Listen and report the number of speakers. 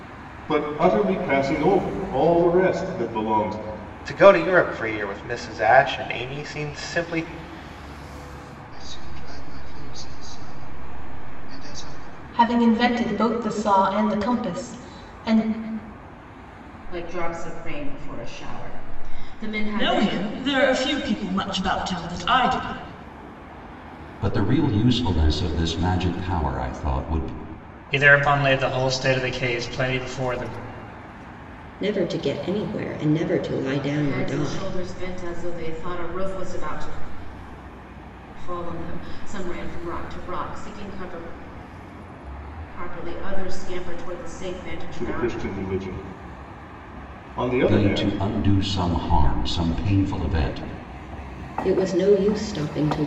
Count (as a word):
nine